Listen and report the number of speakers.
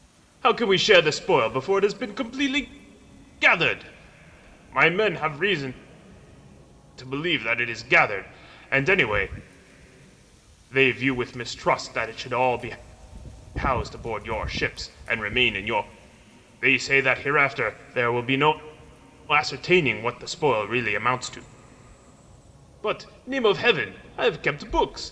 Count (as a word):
one